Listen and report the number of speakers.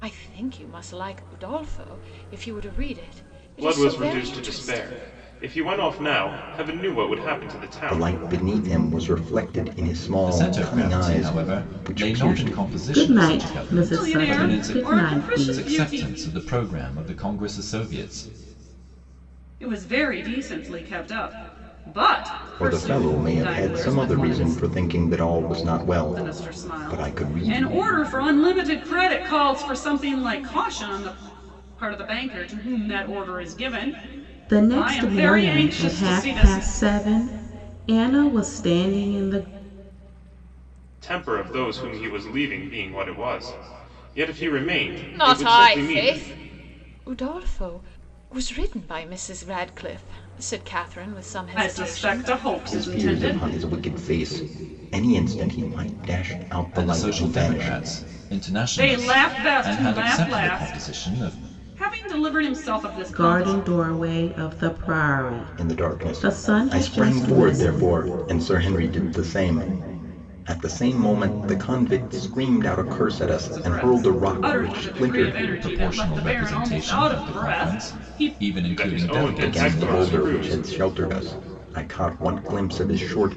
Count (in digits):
6